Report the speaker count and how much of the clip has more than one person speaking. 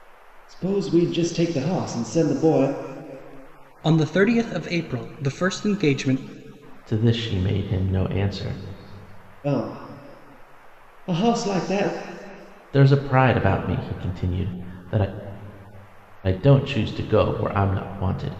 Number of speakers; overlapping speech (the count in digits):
3, no overlap